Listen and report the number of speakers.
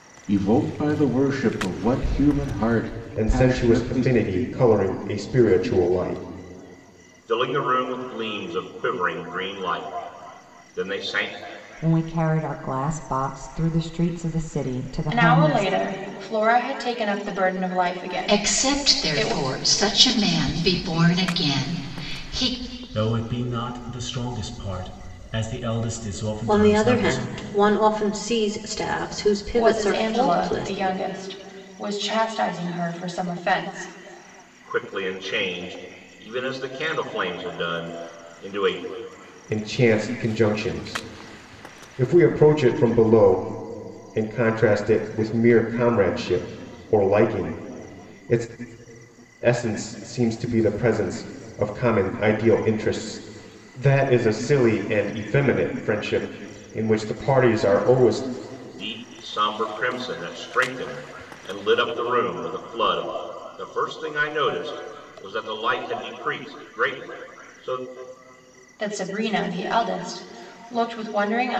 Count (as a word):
eight